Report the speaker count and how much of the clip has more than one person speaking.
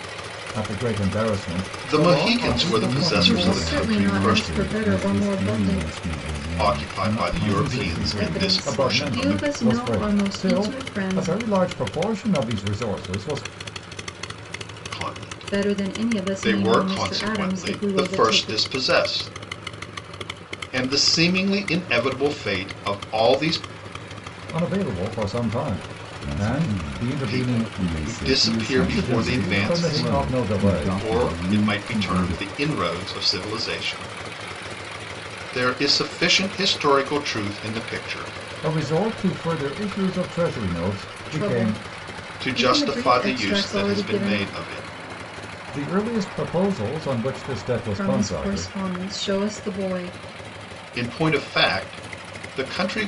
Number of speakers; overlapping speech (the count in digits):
4, about 41%